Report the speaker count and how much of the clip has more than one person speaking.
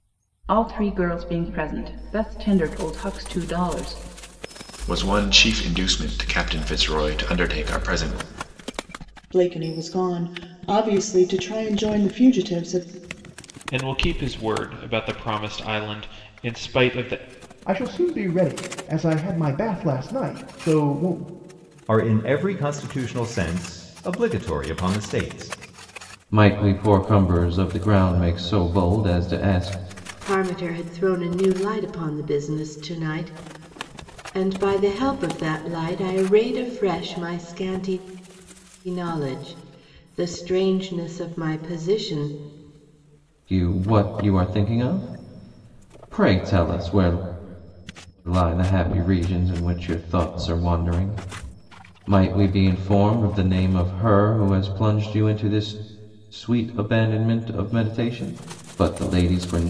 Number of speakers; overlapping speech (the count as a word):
eight, no overlap